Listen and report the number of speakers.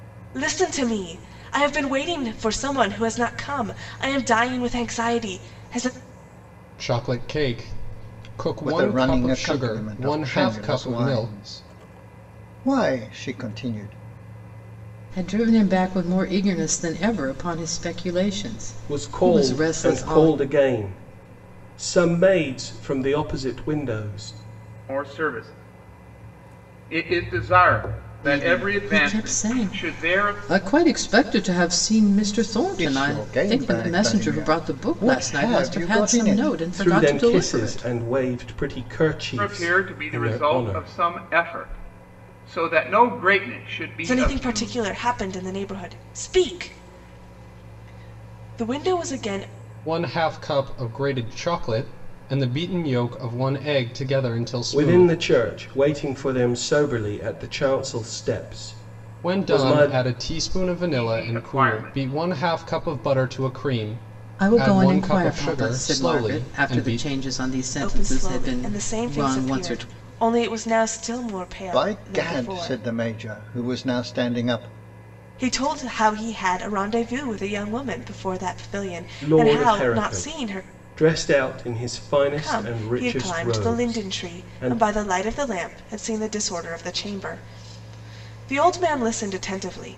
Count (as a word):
six